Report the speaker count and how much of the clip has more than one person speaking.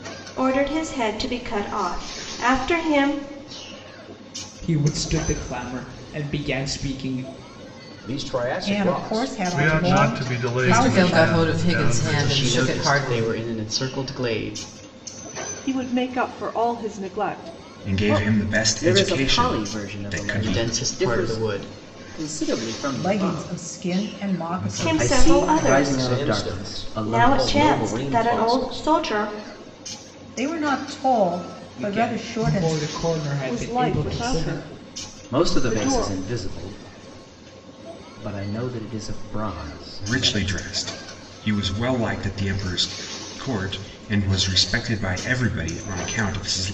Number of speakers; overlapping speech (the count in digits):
10, about 37%